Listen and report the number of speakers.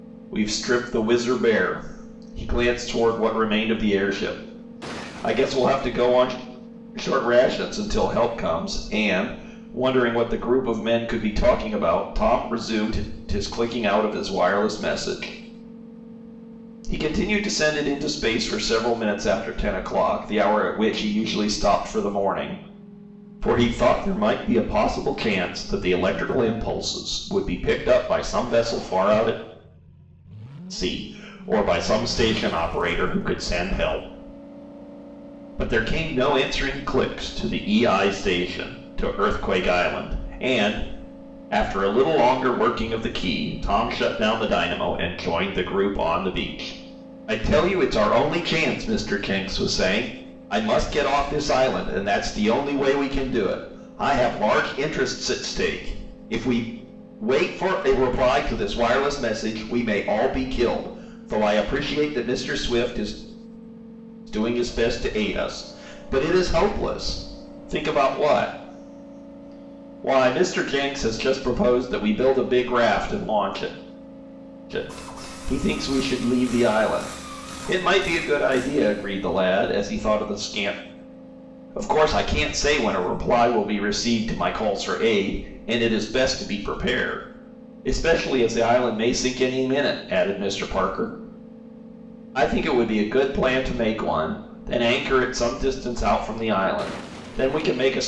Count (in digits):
1